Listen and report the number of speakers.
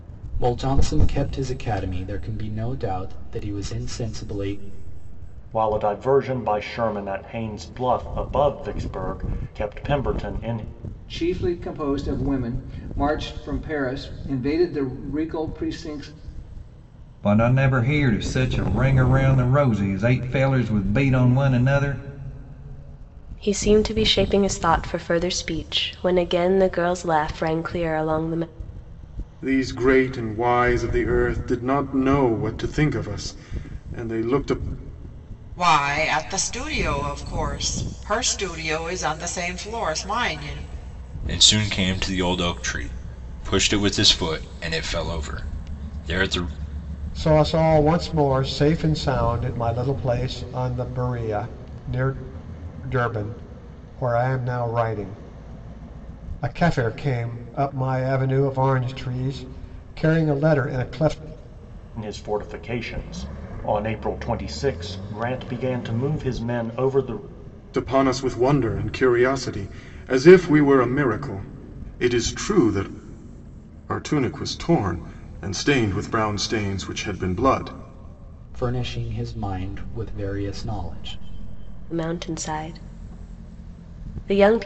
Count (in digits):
9